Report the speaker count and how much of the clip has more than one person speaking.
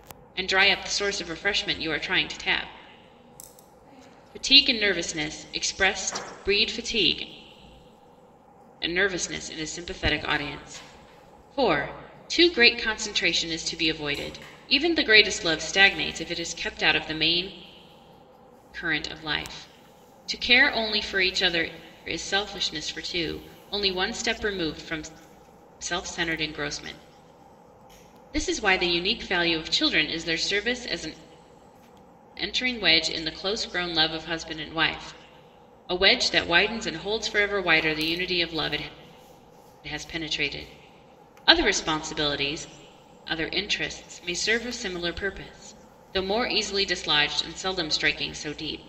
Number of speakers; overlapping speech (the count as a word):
one, no overlap